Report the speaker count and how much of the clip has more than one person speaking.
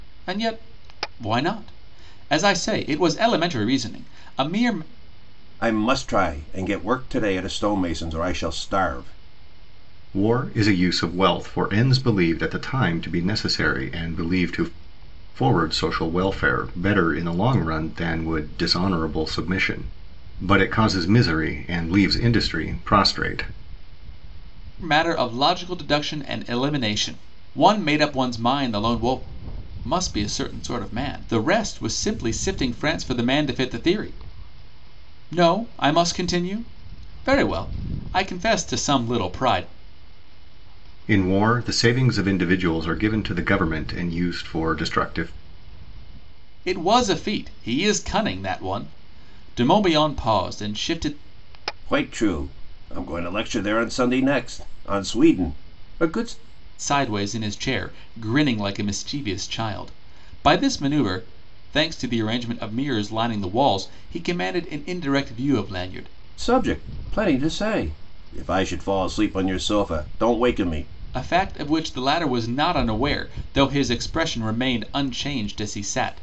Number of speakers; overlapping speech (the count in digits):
3, no overlap